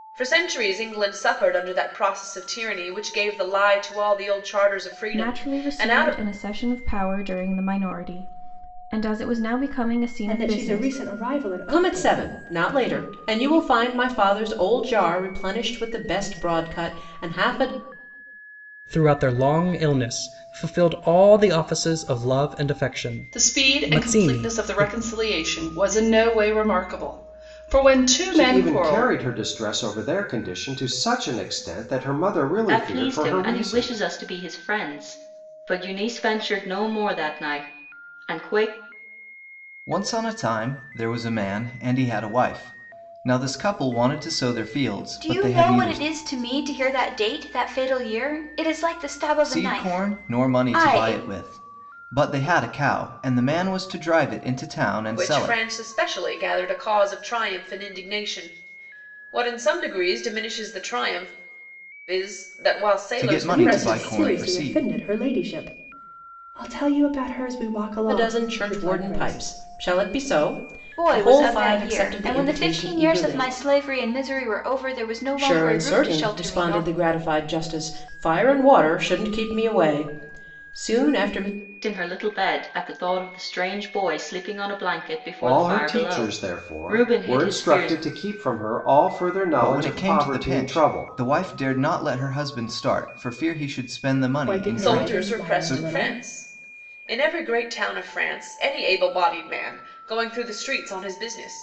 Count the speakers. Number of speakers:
10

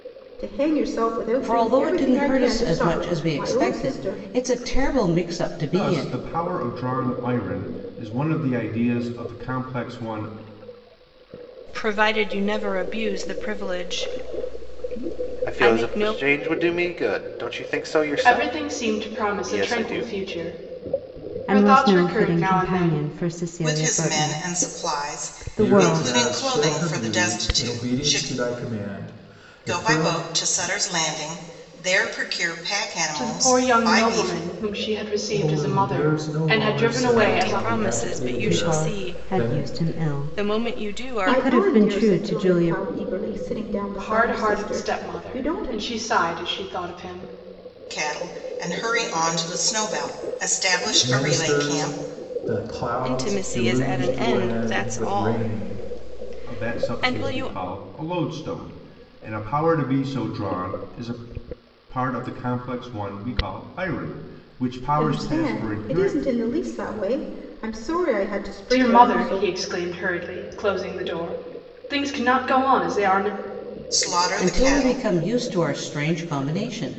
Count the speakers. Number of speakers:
9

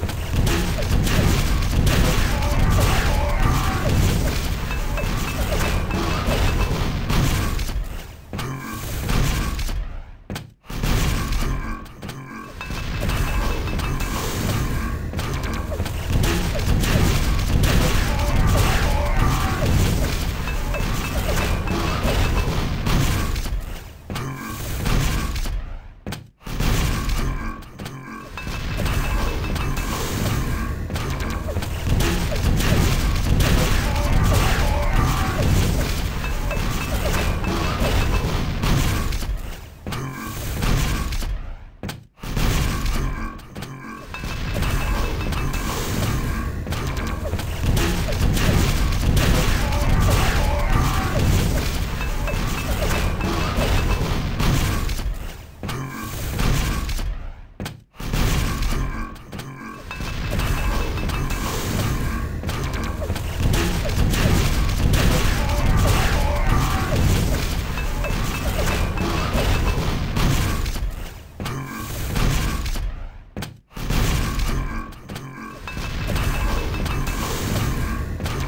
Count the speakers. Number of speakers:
0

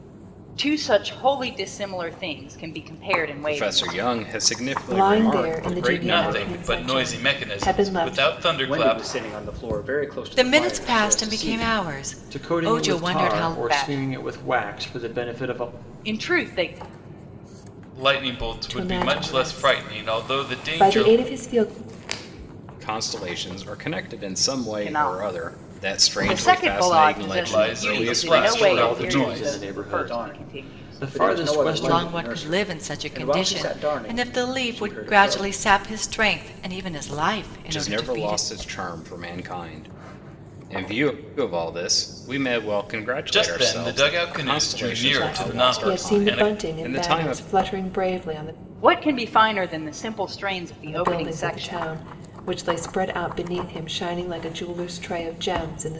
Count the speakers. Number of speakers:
7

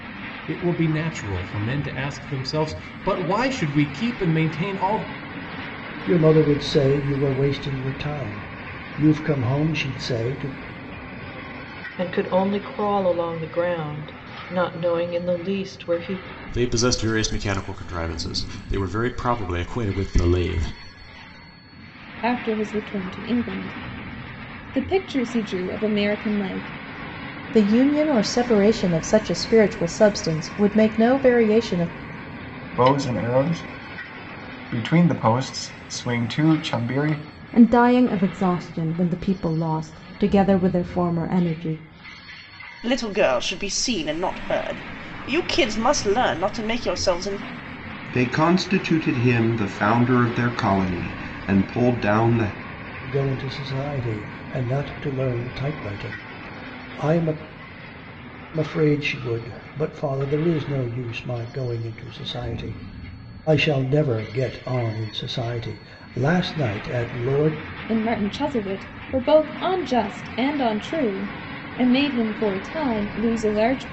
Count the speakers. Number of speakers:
10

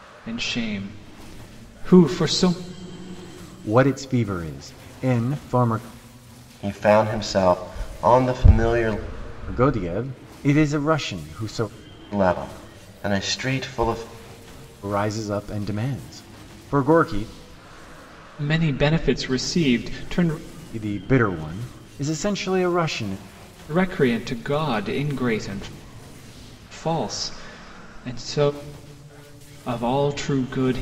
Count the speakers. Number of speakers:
3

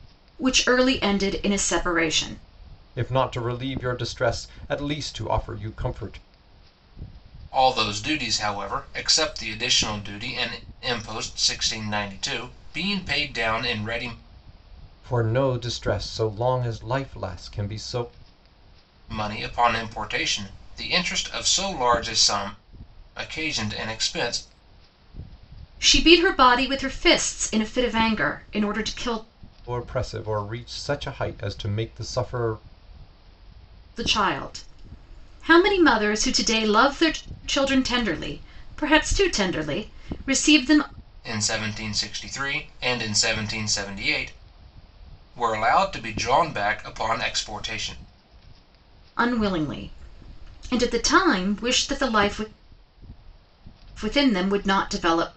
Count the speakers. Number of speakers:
3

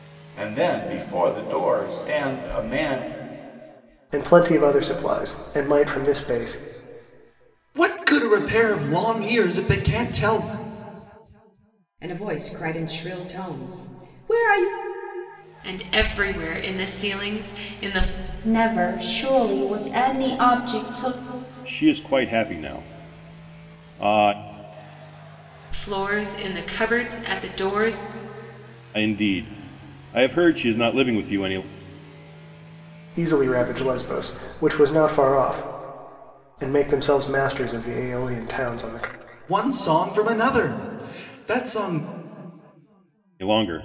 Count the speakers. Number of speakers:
7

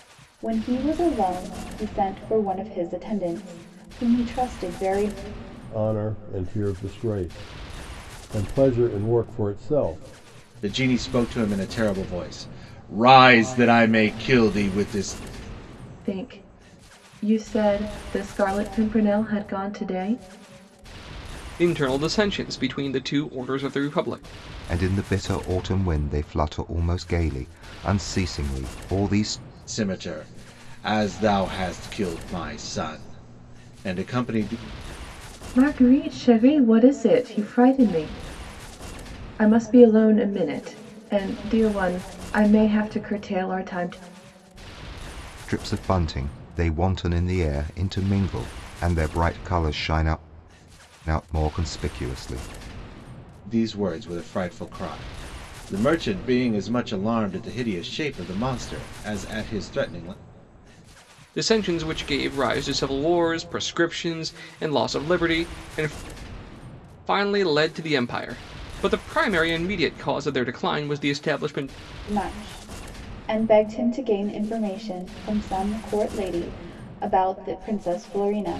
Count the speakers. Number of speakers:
6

